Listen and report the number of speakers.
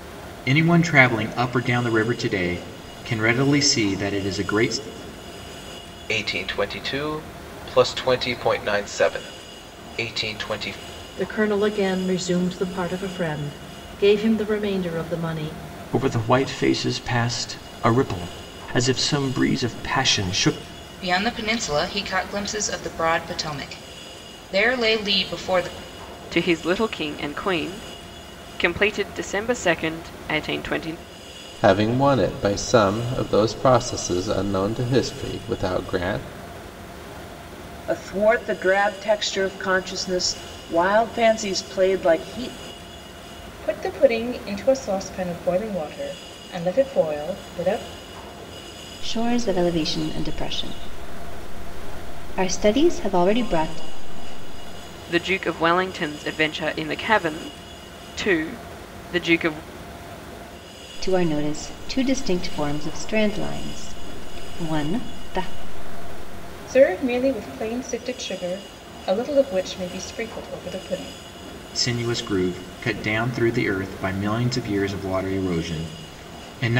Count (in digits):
10